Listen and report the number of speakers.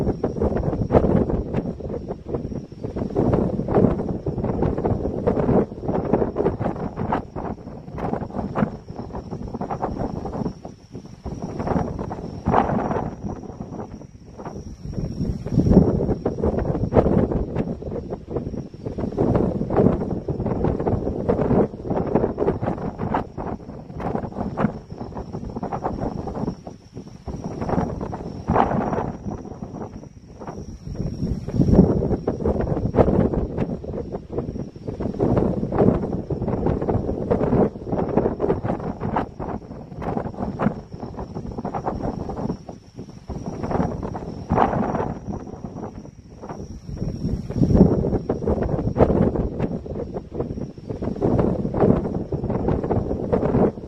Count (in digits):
0